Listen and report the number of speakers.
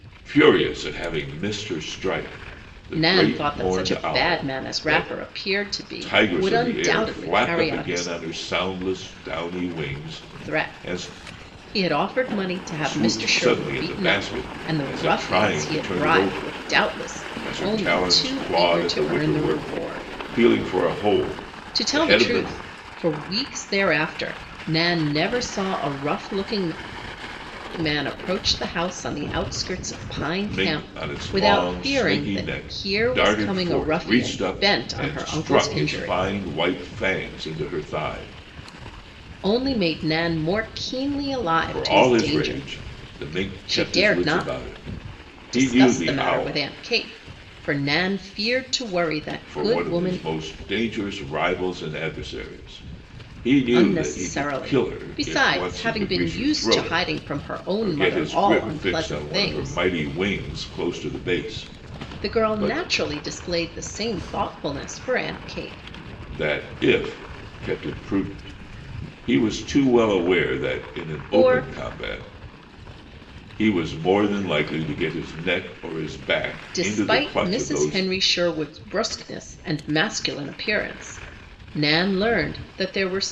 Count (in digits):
2